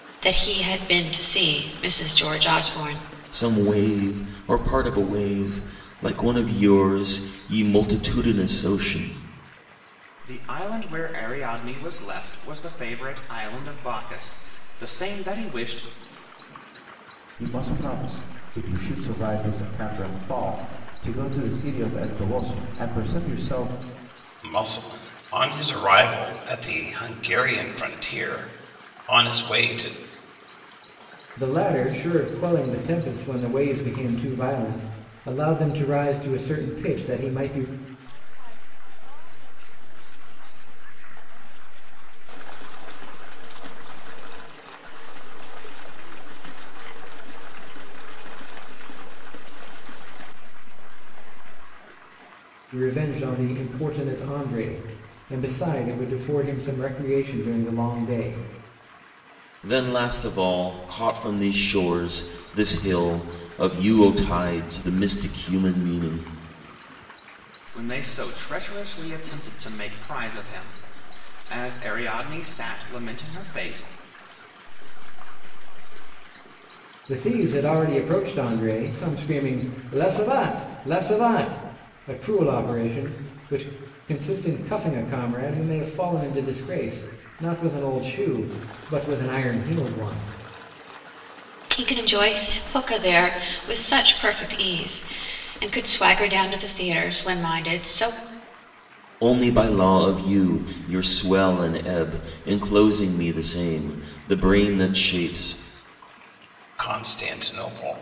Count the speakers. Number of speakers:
7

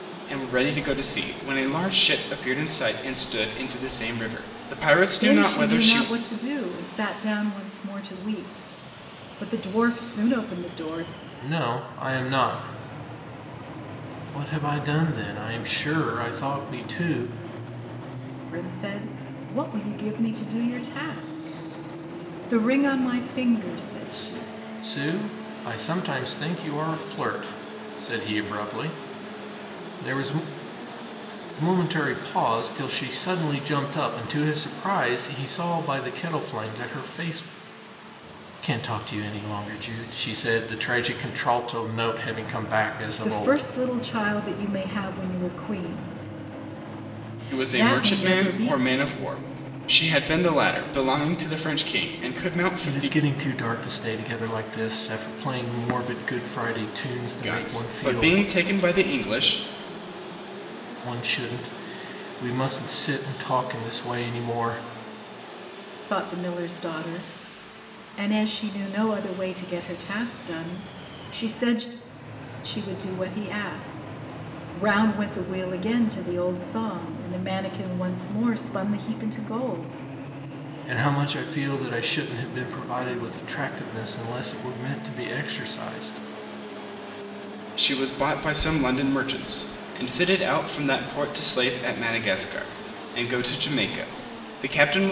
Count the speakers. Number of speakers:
3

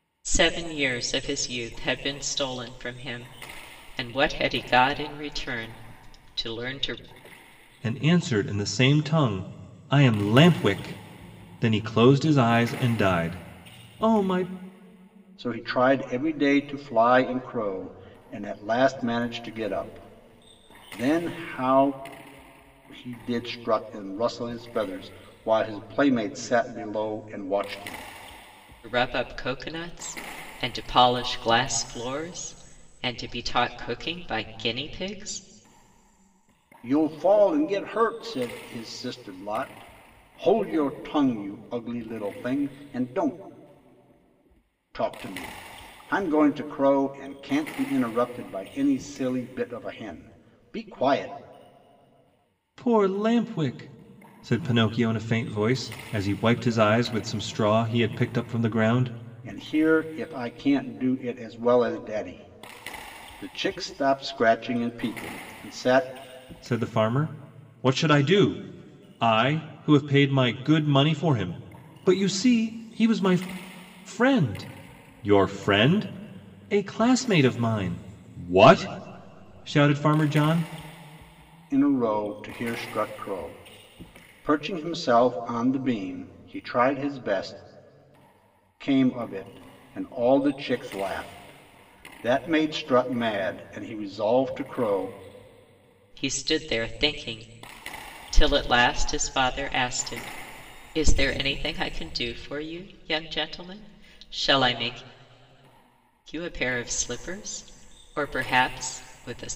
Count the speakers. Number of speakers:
3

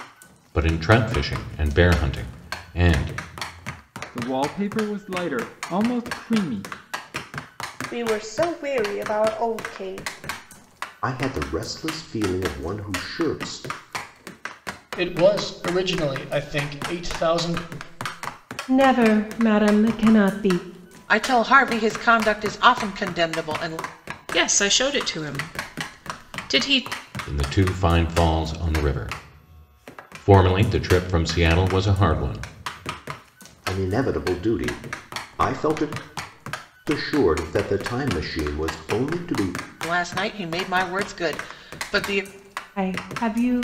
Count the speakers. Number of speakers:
8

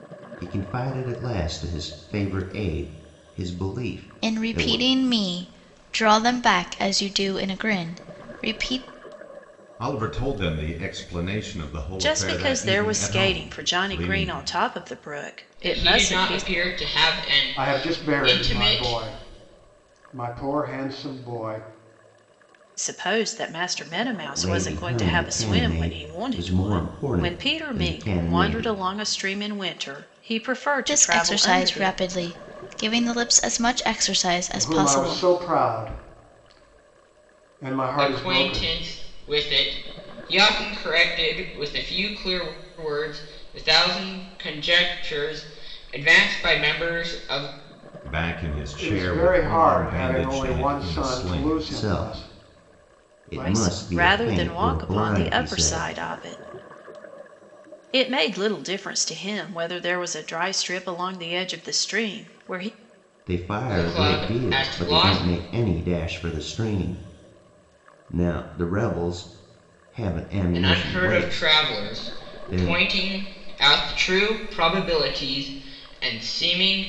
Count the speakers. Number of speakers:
6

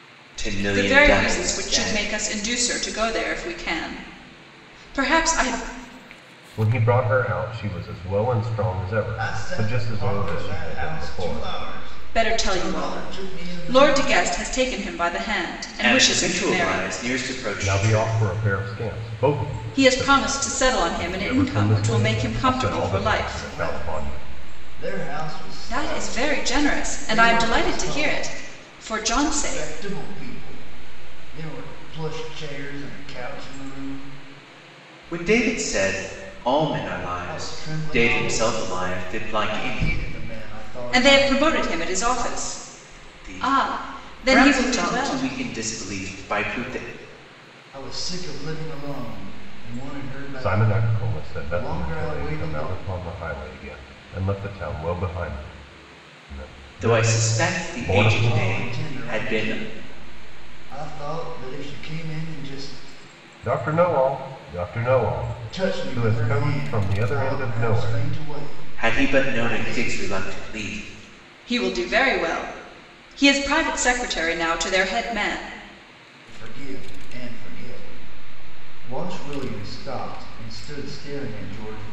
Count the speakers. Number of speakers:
4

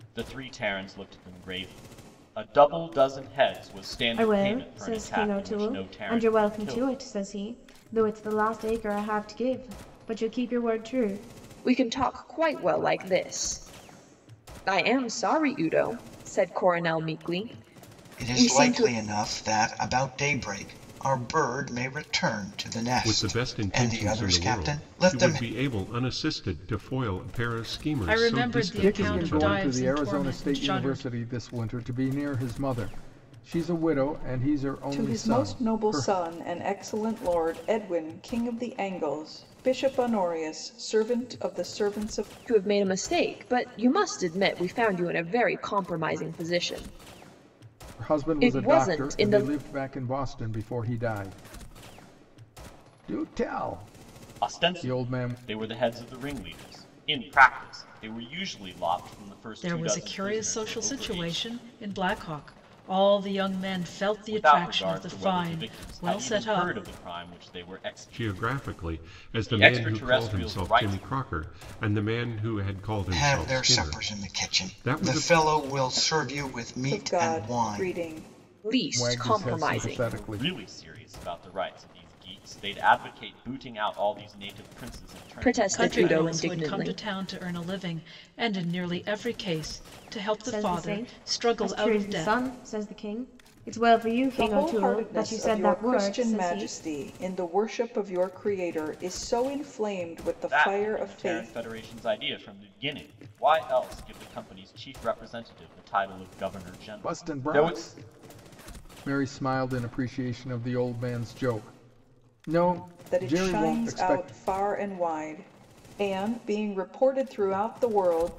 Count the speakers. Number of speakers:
8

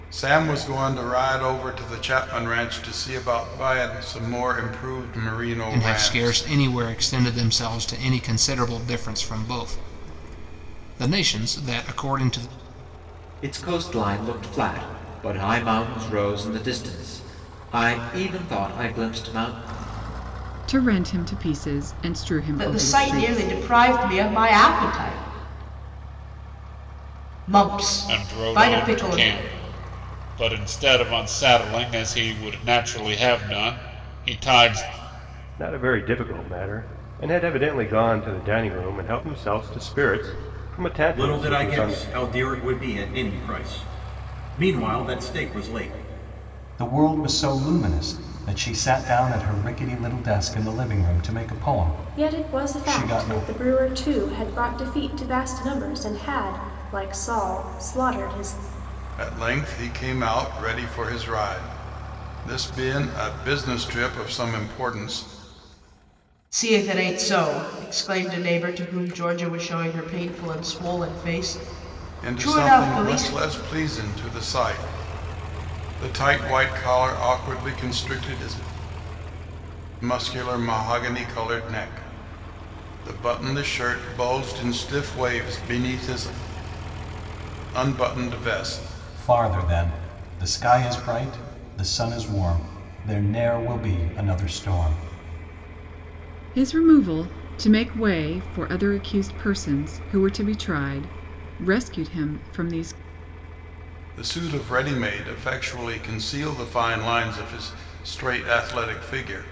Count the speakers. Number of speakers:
10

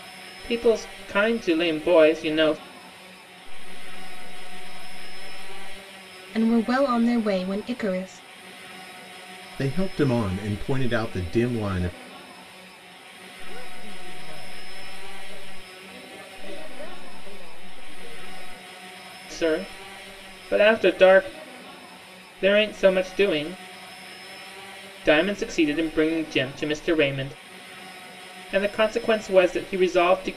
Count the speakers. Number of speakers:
5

